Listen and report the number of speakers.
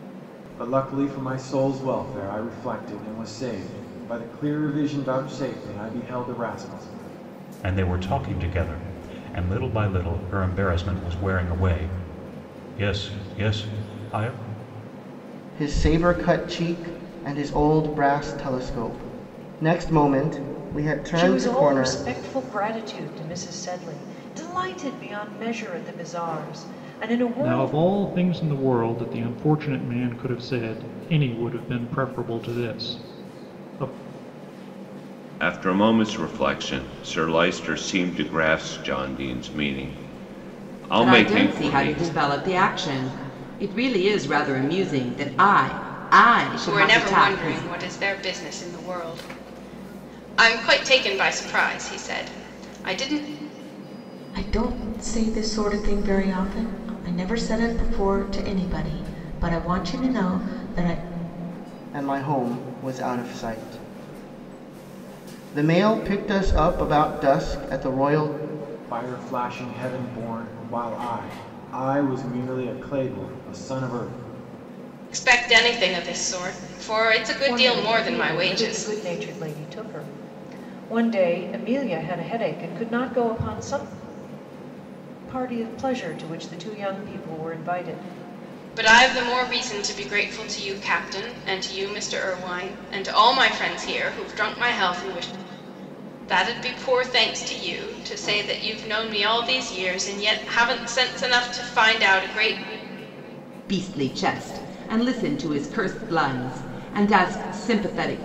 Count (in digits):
9